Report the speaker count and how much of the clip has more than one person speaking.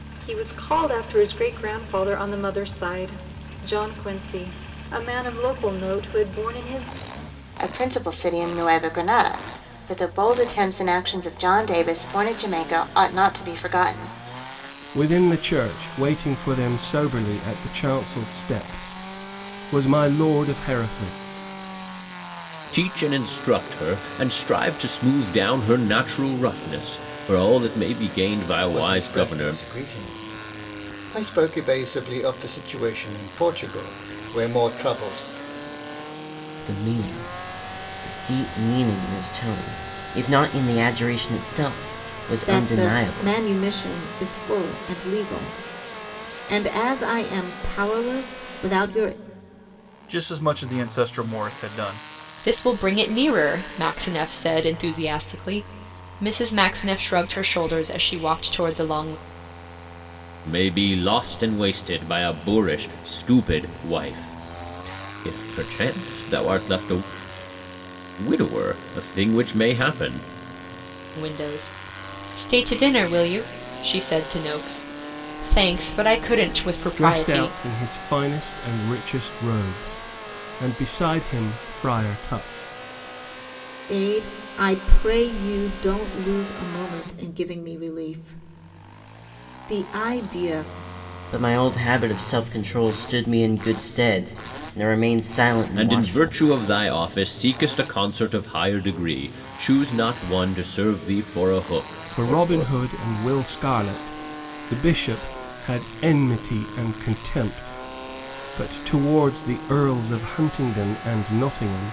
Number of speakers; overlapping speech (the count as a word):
nine, about 3%